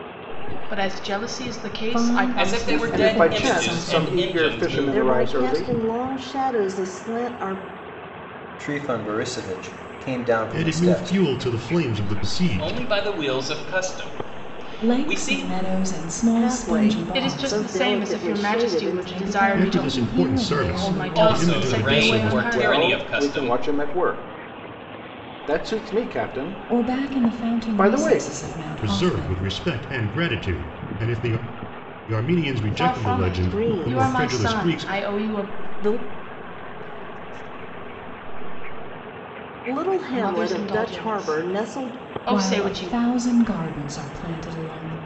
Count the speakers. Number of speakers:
8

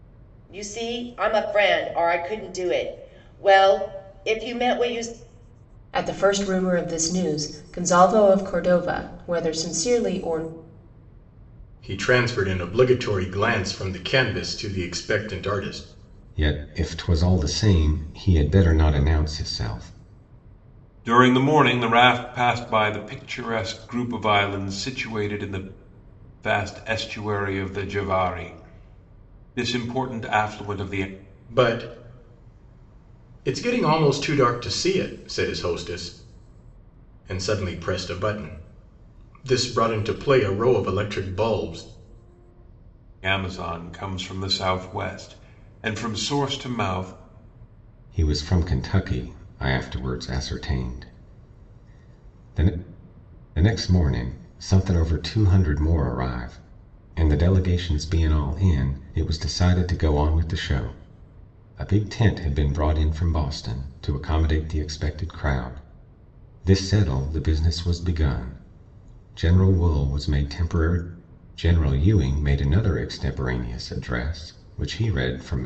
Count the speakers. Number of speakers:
5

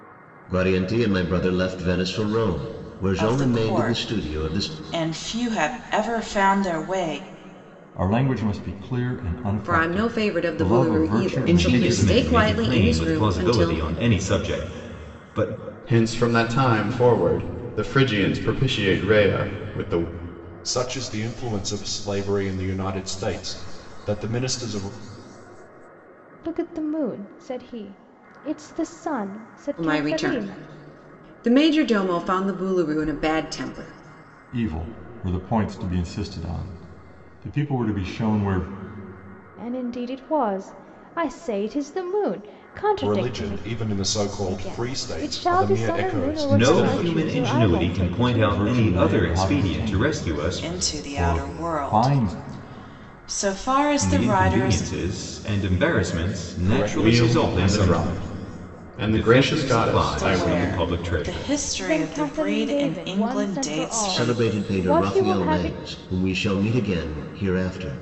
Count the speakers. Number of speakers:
8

